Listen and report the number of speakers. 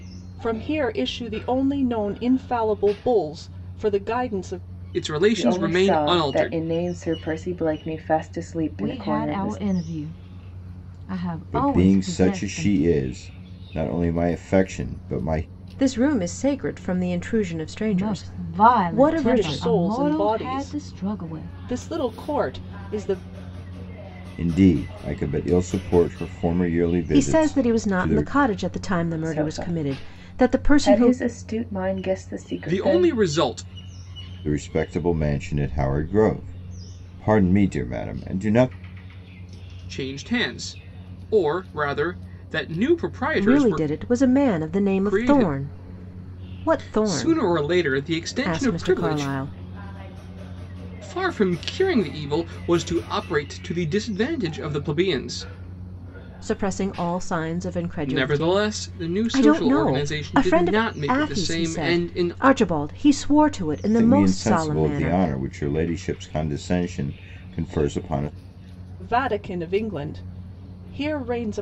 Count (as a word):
six